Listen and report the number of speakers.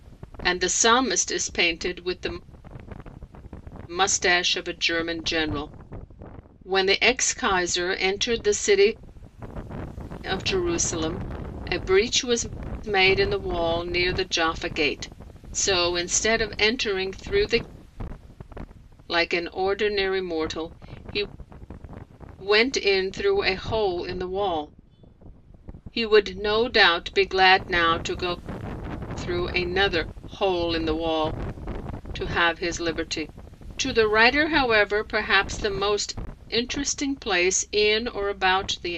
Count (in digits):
1